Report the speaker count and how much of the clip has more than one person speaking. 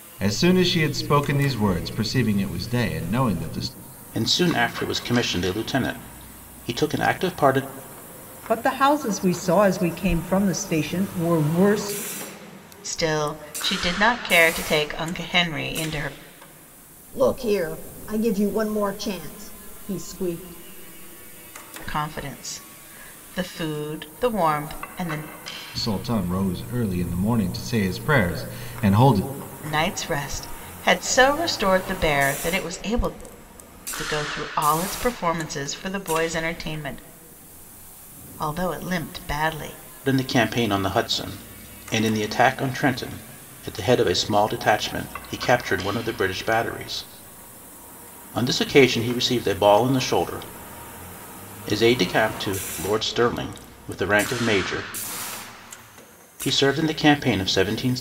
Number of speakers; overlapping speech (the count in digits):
5, no overlap